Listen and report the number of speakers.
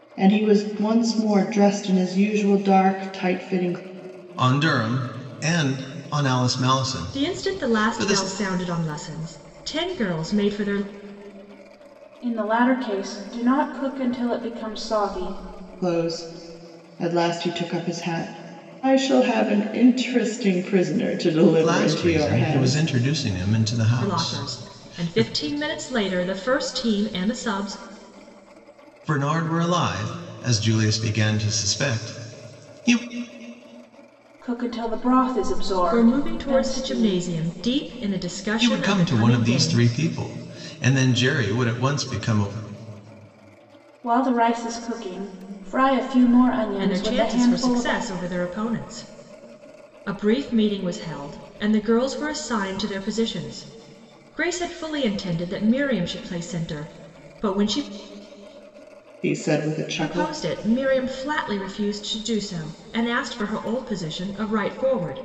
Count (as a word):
four